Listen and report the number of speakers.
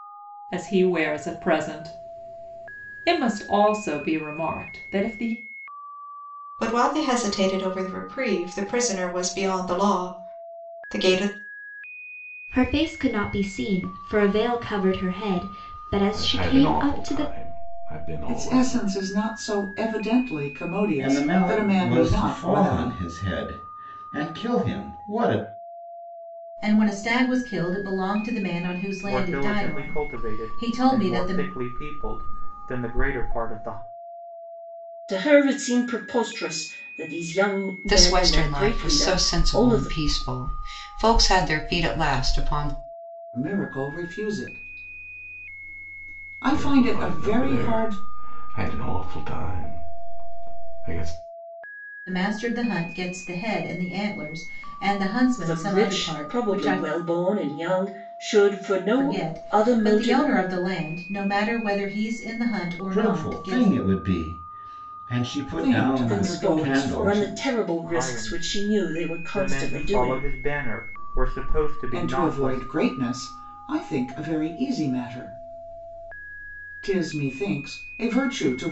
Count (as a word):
ten